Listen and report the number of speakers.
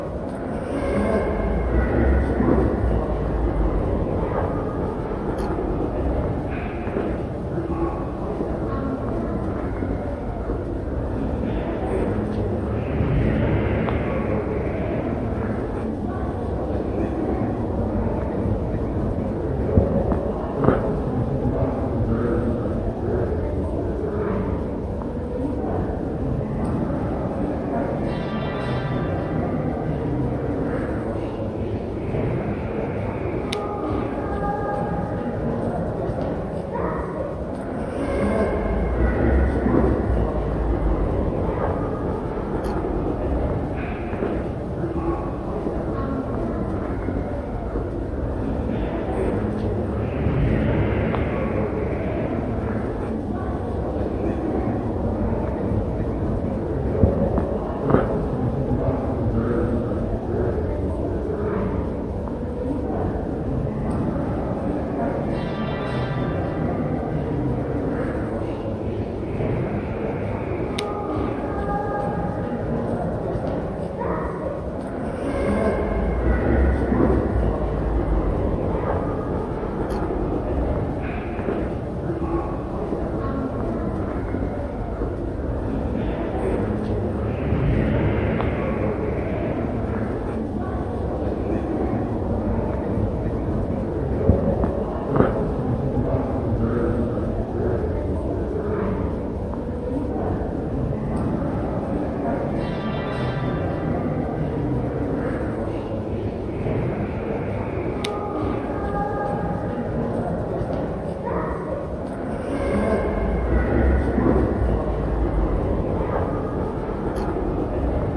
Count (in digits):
0